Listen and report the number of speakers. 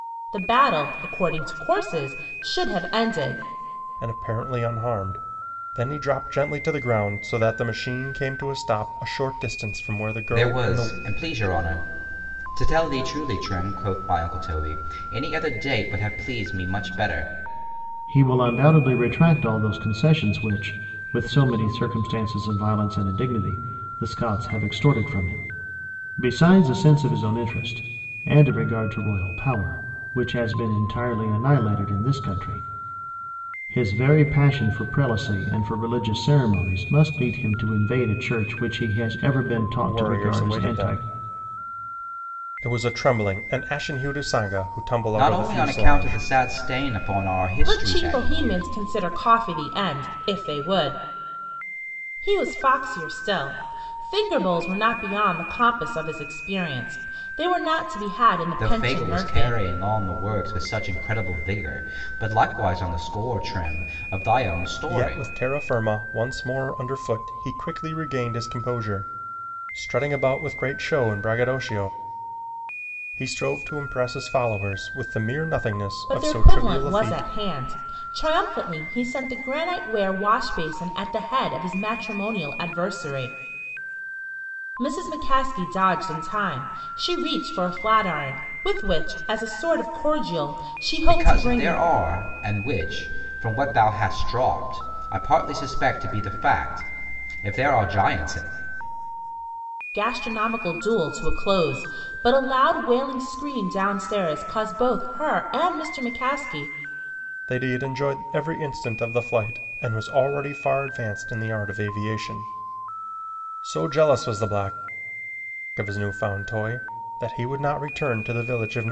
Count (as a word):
four